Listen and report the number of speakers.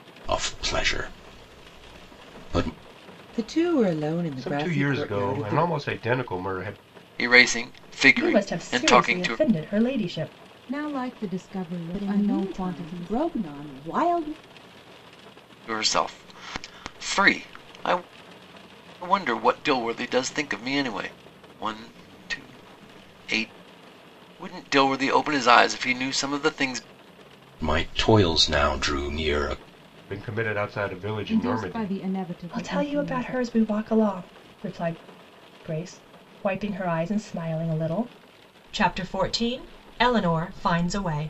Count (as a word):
seven